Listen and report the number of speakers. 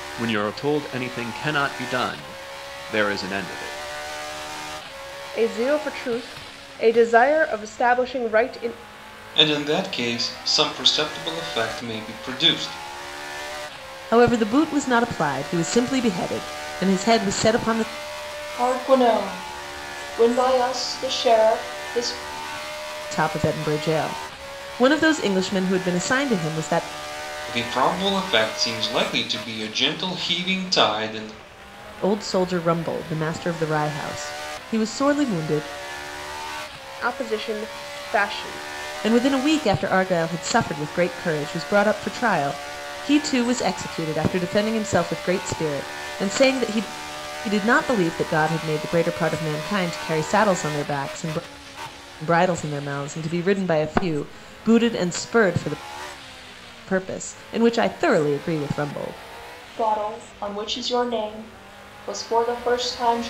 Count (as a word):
five